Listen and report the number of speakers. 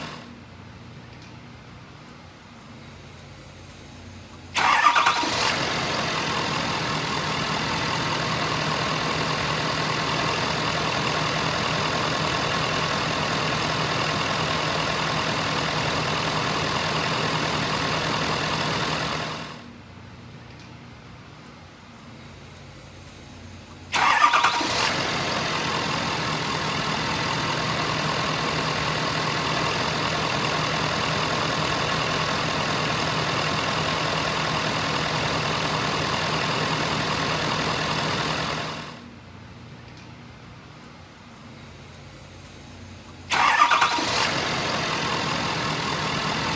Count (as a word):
zero